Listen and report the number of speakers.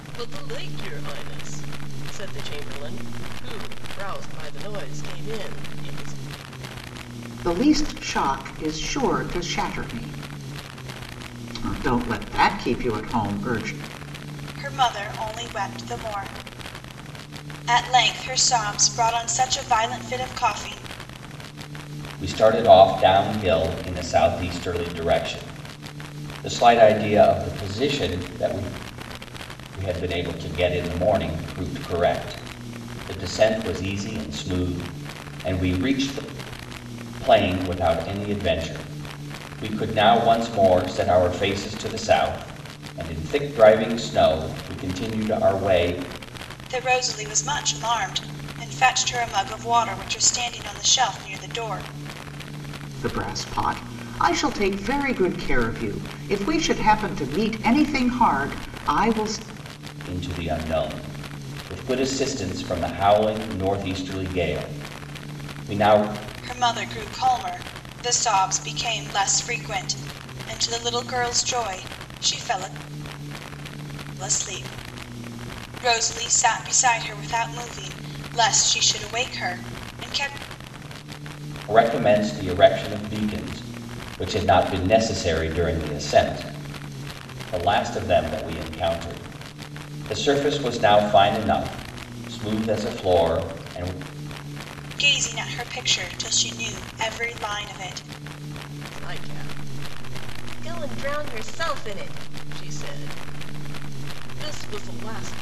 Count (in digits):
4